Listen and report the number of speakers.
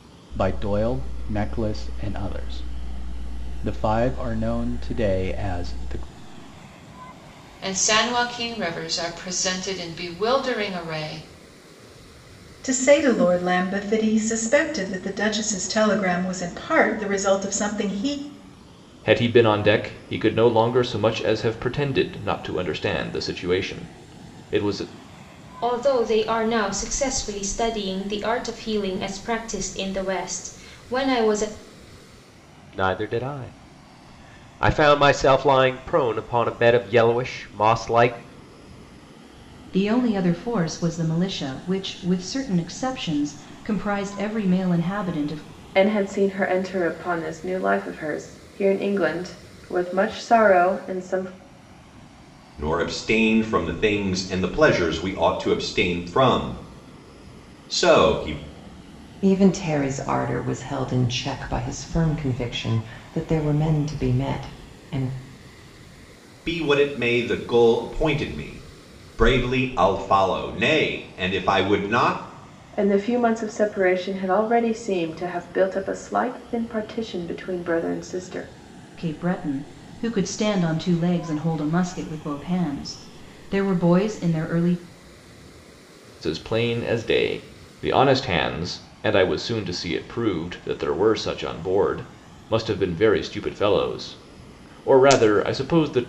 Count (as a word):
ten